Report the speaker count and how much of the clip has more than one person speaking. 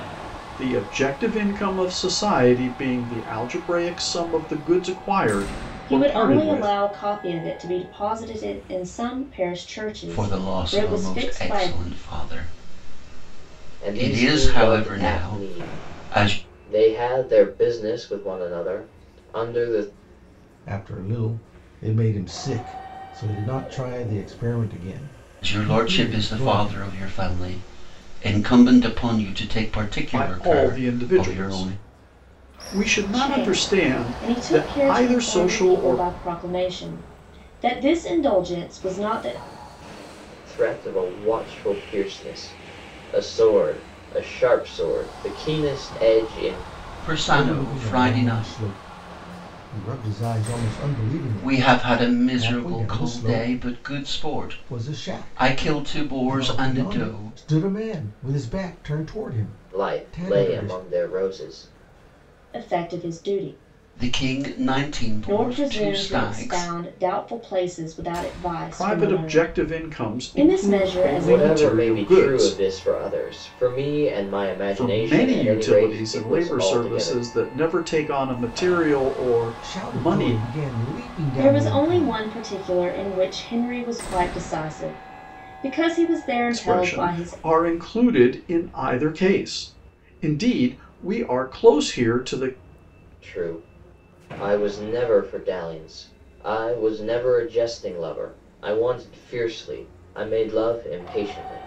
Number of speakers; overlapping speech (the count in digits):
5, about 29%